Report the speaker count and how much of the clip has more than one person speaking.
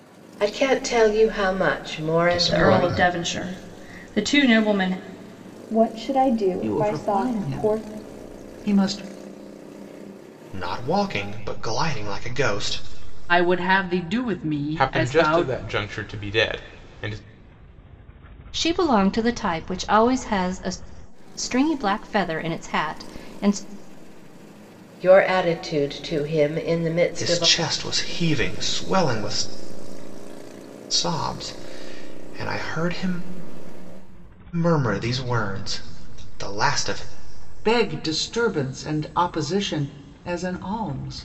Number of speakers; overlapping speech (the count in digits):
9, about 8%